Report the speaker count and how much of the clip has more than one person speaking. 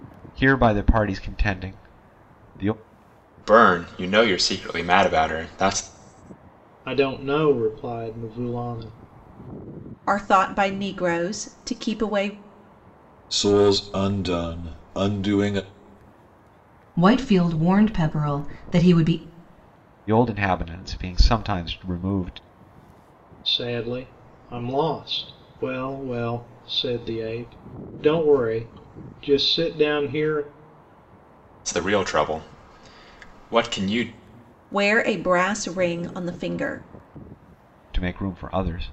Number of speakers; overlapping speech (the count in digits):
6, no overlap